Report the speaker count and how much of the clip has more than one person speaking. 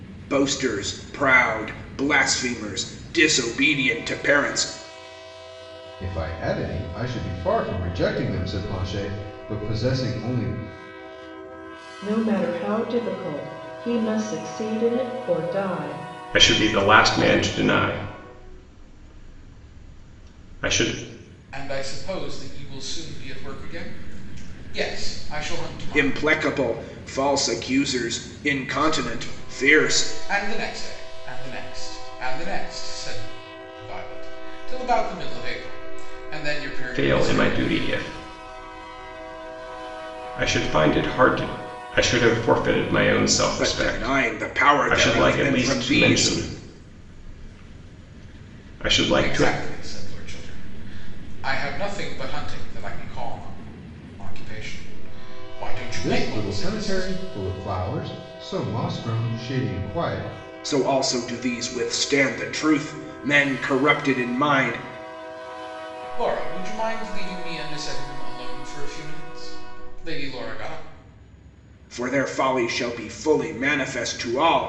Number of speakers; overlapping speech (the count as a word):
five, about 9%